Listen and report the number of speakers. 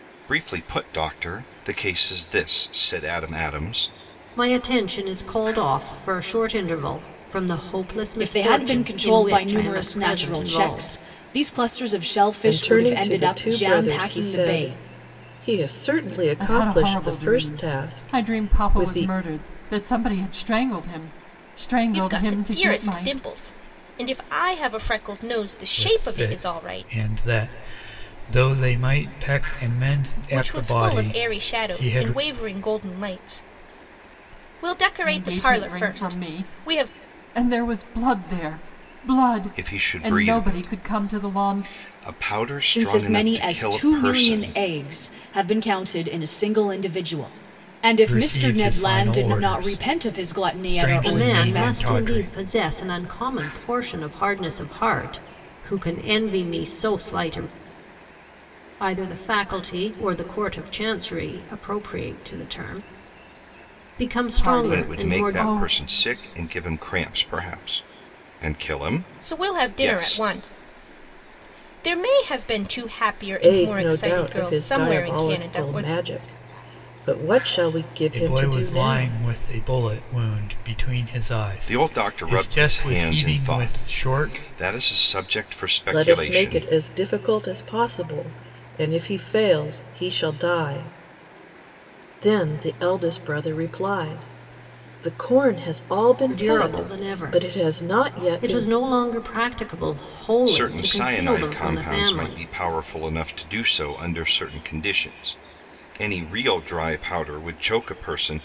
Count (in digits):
7